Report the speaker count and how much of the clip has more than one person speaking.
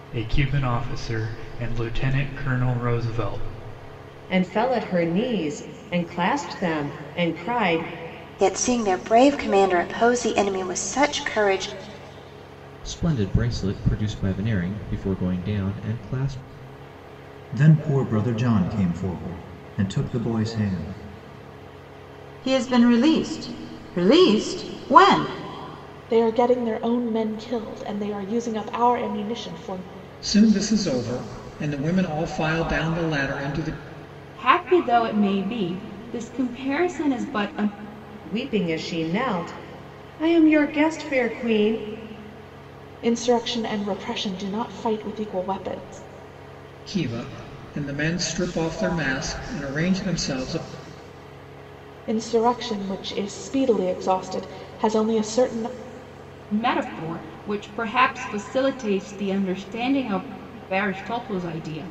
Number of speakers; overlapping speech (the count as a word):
nine, no overlap